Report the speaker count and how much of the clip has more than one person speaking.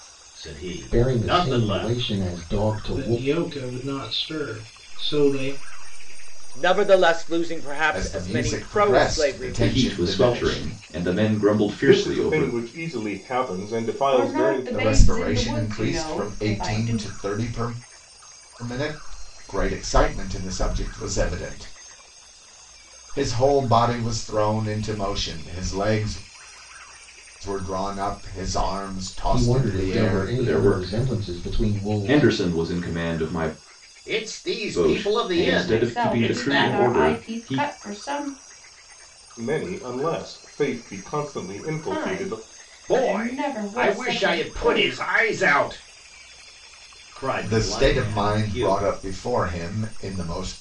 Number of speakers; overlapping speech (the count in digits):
9, about 40%